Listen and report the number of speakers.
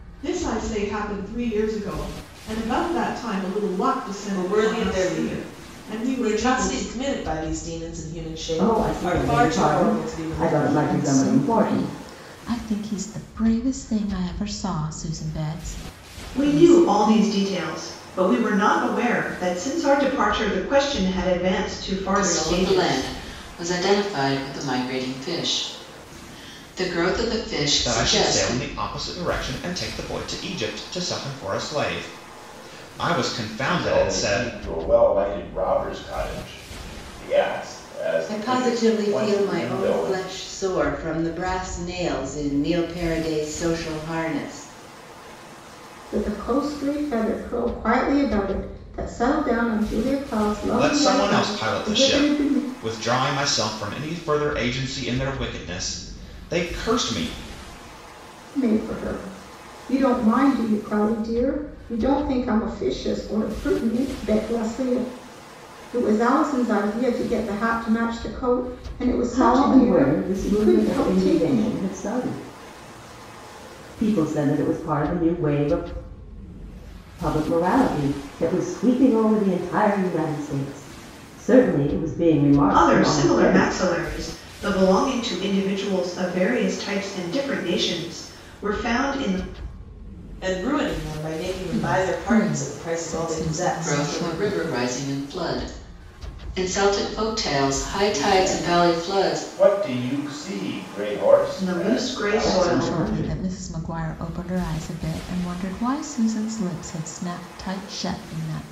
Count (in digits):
10